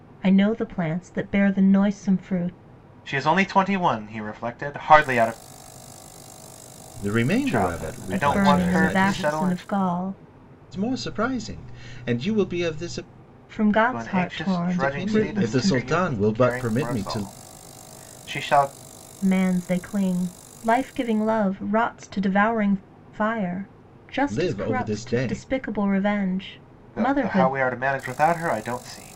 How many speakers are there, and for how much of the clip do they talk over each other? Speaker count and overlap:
three, about 26%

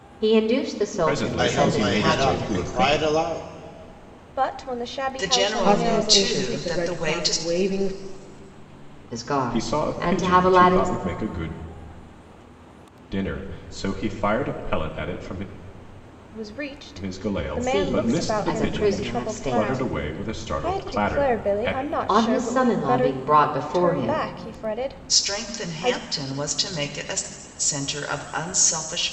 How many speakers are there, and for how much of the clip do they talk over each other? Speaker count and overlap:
six, about 46%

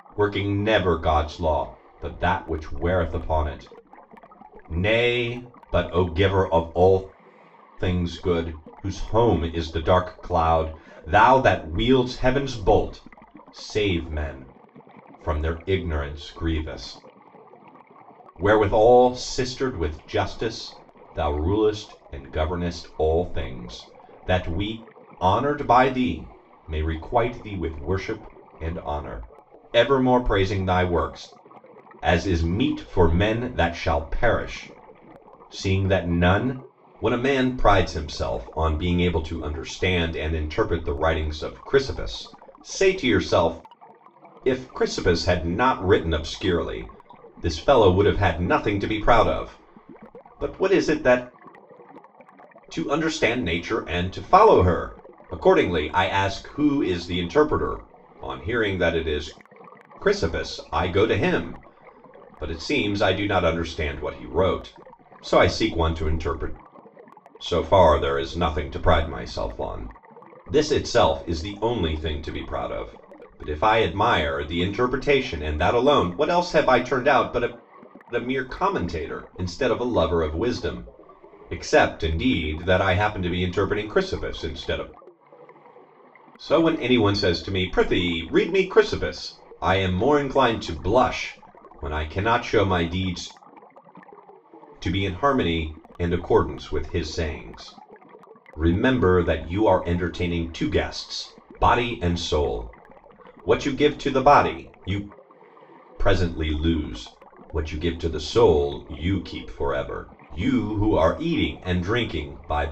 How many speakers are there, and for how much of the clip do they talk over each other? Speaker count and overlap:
one, no overlap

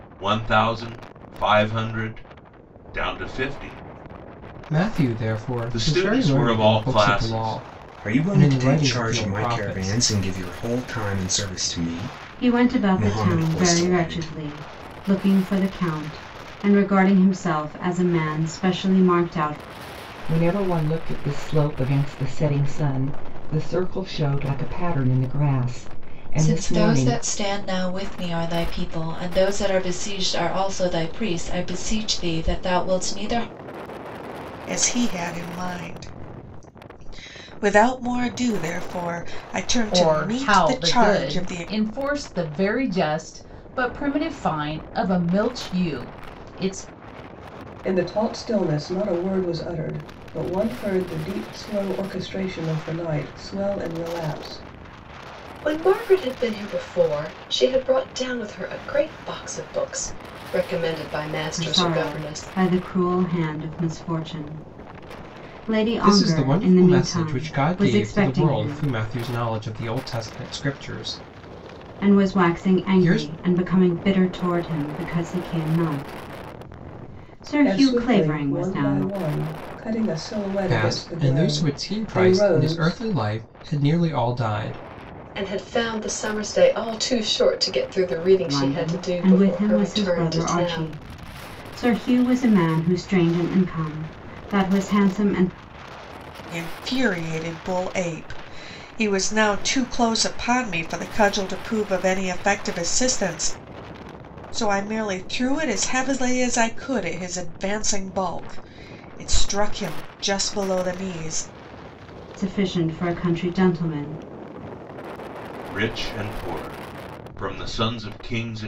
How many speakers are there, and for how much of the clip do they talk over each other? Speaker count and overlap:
ten, about 18%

